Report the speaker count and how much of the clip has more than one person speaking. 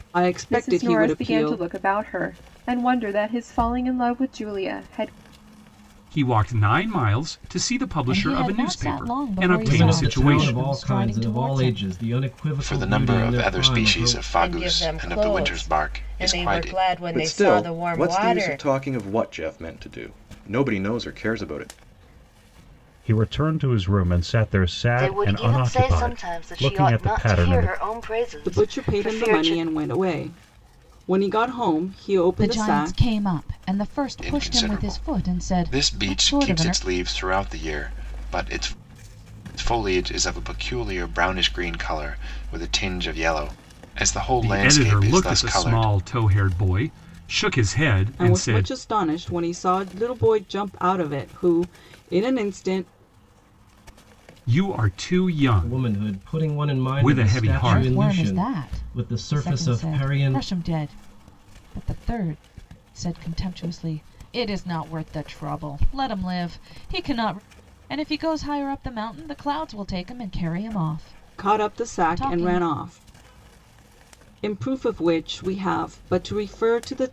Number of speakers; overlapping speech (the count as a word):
ten, about 34%